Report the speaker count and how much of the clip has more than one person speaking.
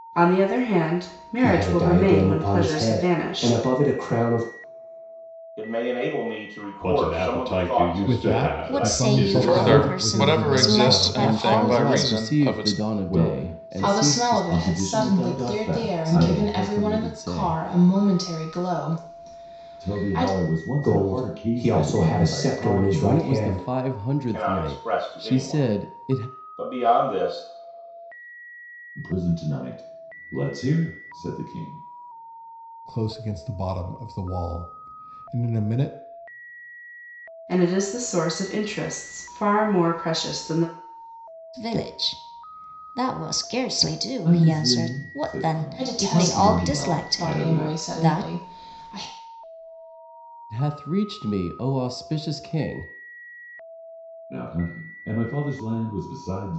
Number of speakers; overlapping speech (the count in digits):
10, about 40%